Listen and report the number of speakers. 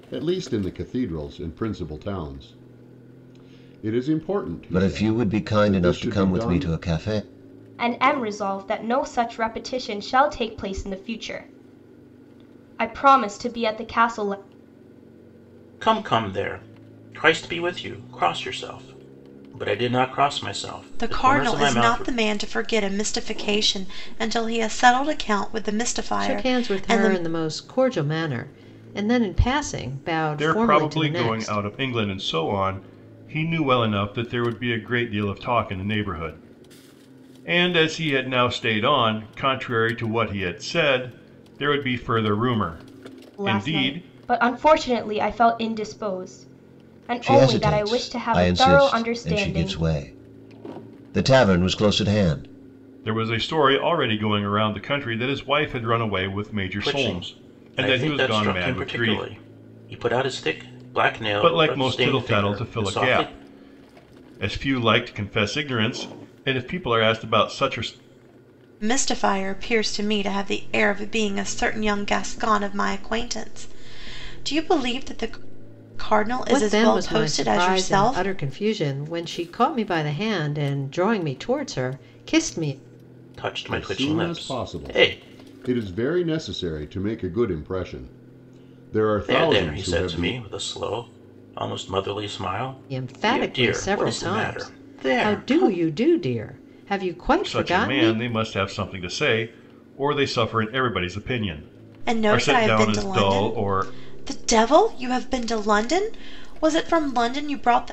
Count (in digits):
7